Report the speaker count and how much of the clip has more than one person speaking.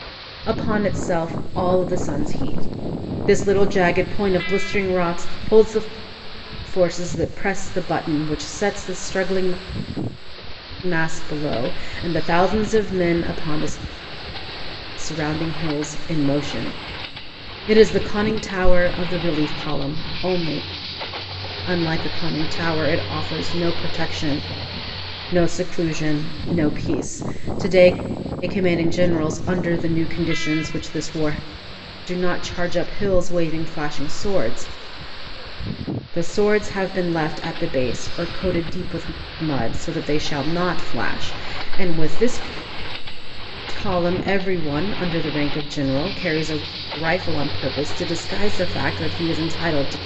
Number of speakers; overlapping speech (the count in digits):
1, no overlap